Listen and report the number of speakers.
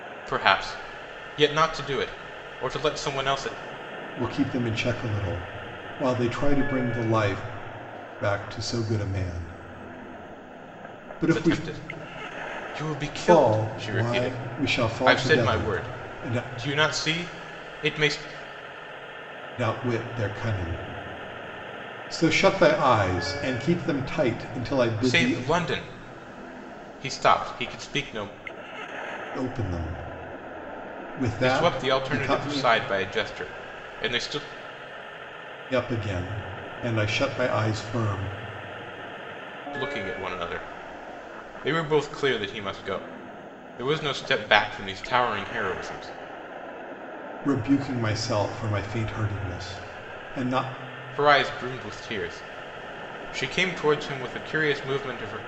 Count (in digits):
2